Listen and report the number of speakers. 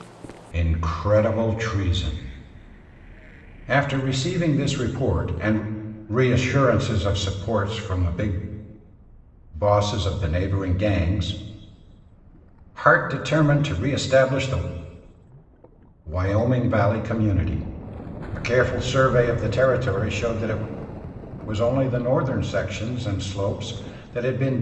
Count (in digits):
1